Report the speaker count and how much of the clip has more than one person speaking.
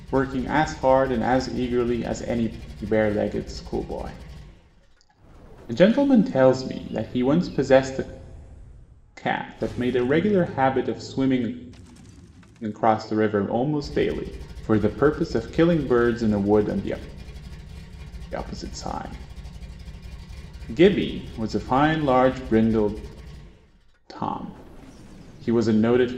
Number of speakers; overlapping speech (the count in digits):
1, no overlap